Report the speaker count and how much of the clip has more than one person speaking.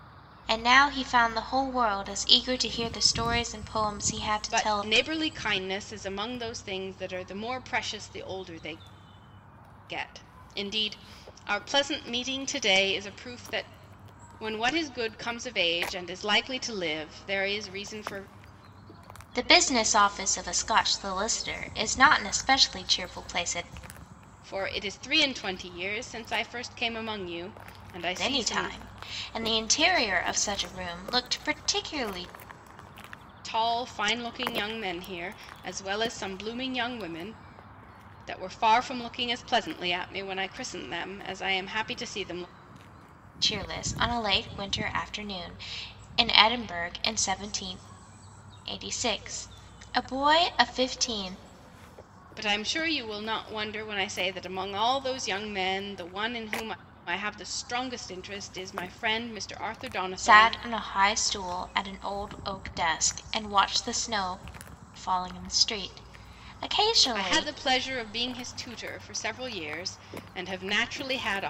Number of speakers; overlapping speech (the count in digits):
2, about 3%